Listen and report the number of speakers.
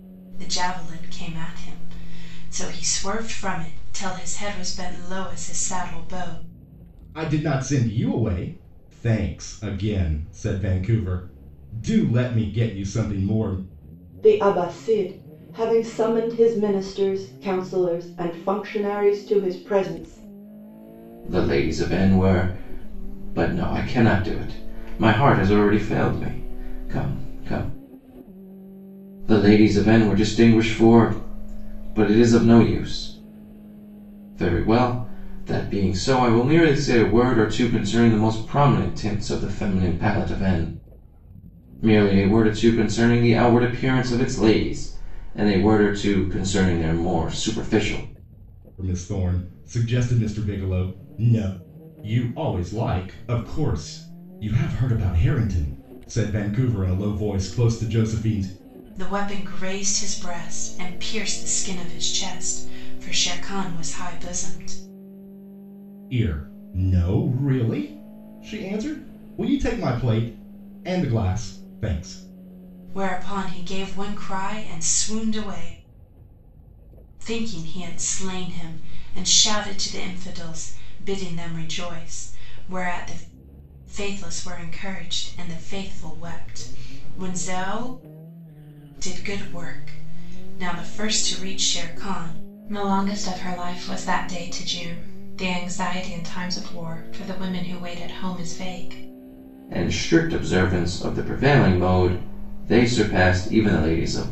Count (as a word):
four